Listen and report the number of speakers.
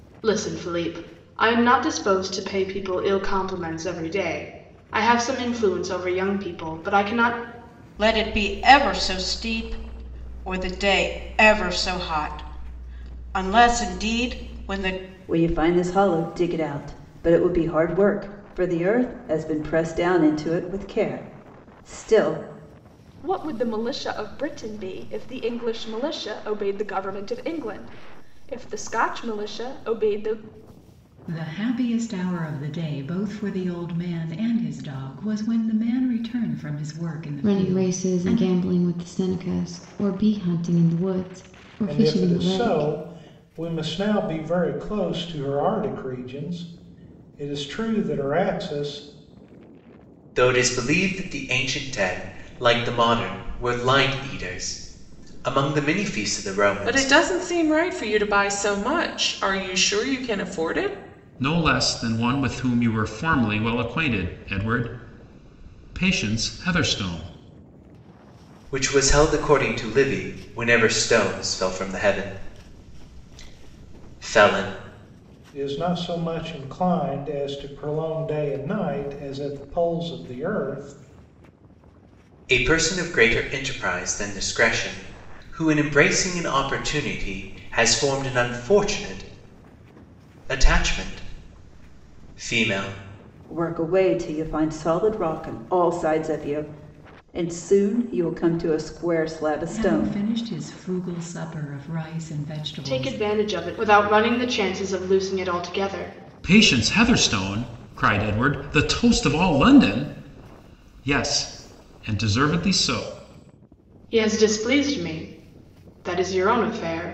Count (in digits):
10